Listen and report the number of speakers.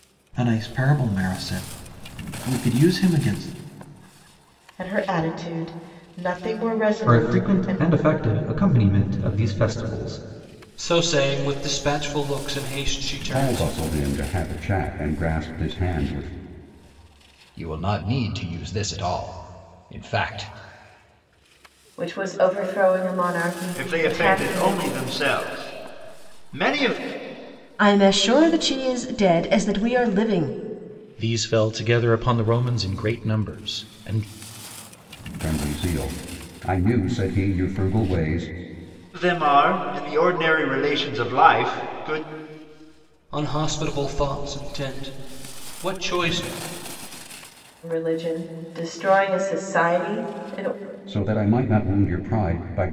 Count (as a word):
ten